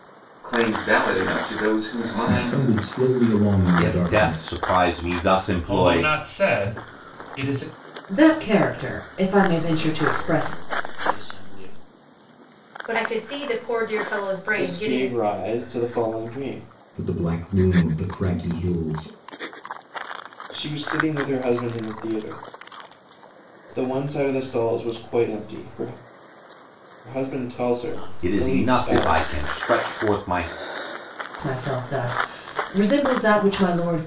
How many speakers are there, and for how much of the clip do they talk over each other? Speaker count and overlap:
8, about 15%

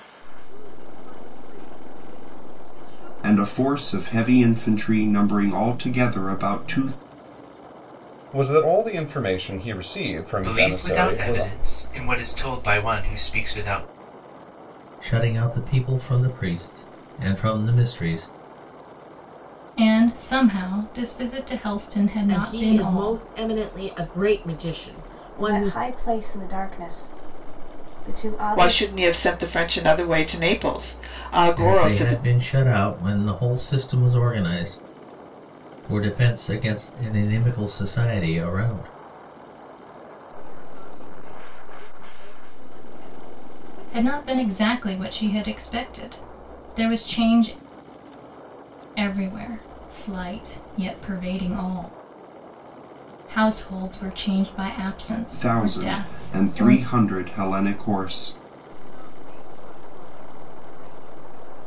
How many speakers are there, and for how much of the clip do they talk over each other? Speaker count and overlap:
9, about 10%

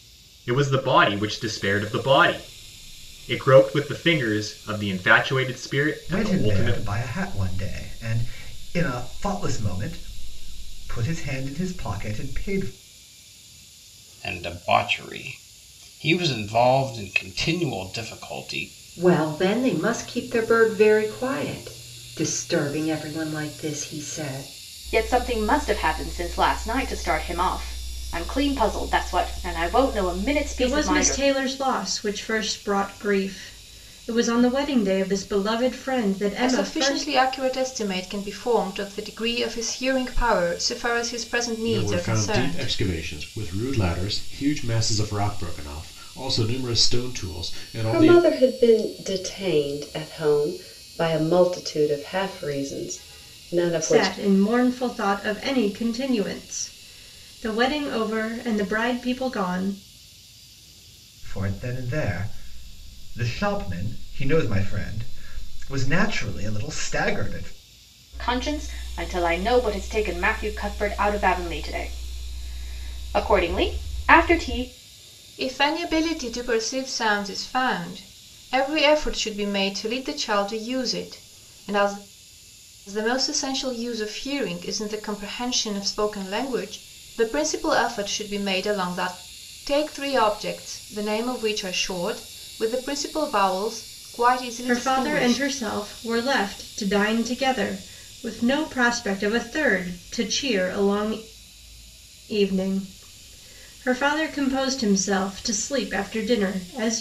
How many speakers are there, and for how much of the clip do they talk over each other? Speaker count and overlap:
9, about 5%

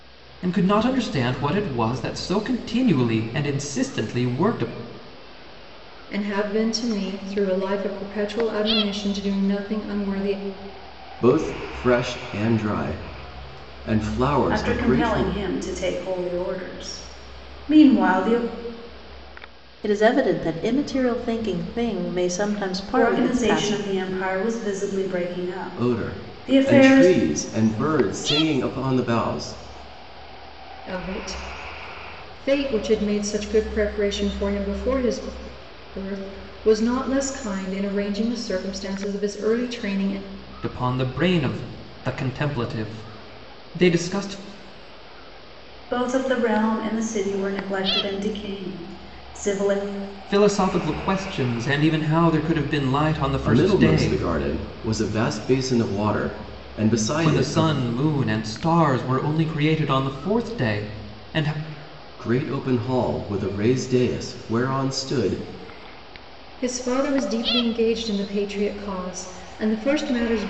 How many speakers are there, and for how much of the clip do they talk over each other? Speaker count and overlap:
5, about 6%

